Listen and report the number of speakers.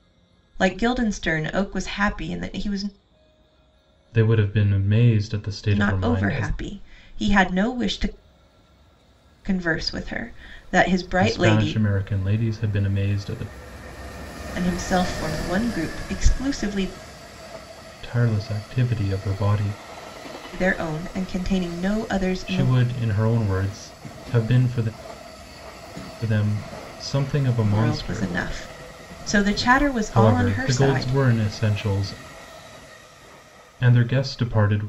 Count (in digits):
2